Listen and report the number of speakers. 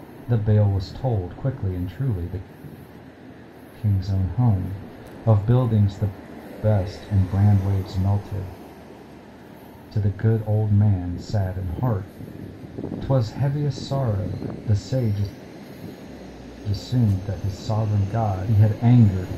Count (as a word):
one